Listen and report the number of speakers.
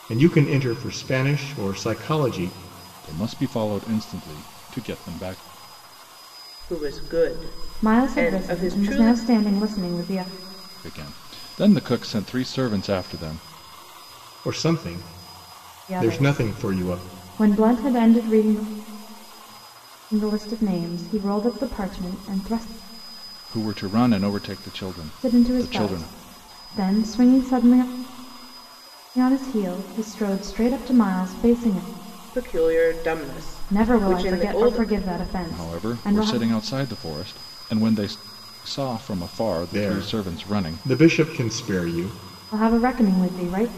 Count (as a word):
four